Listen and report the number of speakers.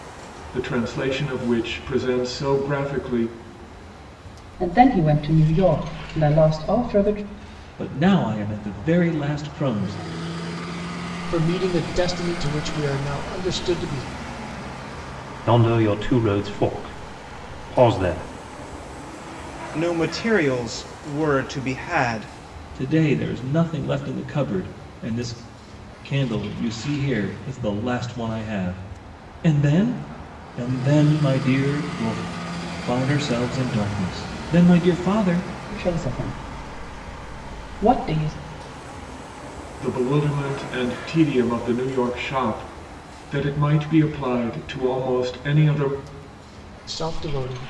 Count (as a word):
six